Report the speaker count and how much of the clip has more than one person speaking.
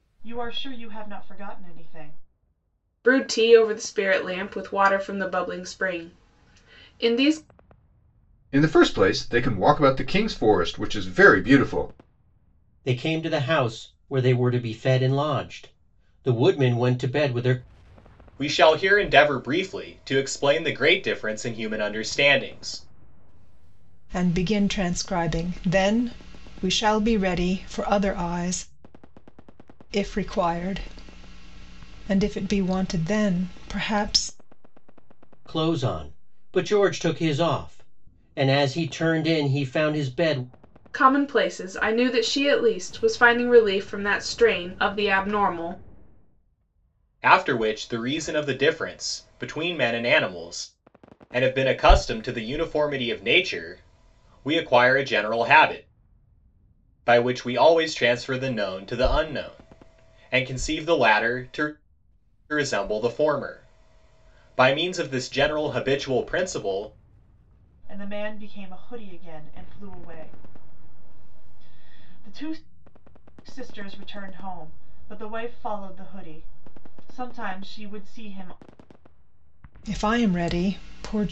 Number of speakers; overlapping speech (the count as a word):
six, no overlap